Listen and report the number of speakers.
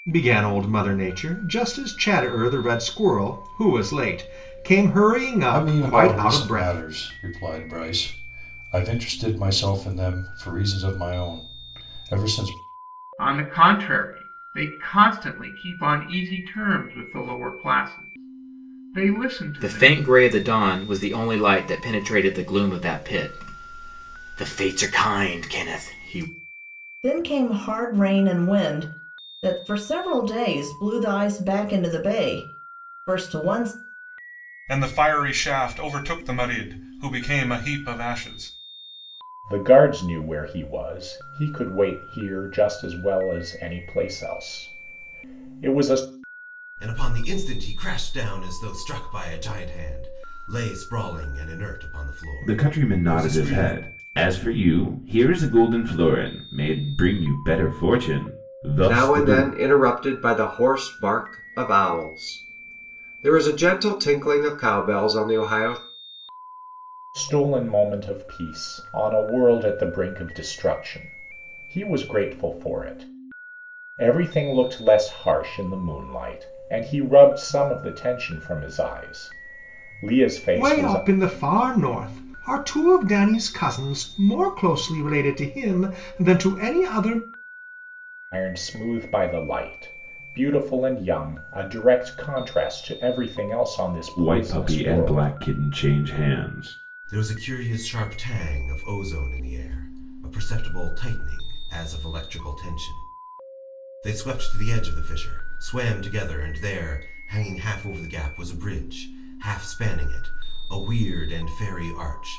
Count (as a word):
ten